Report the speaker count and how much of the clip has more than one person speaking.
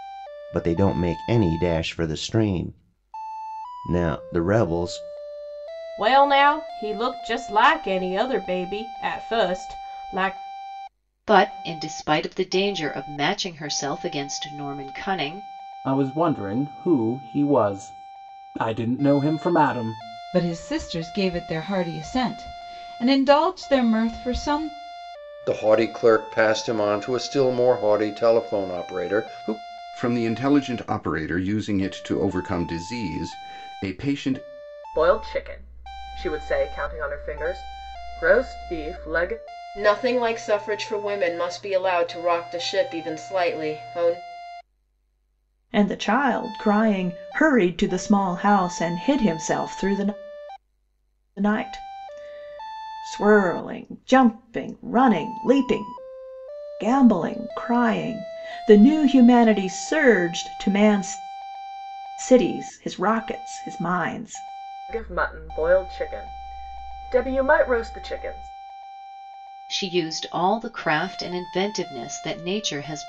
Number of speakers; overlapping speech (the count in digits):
10, no overlap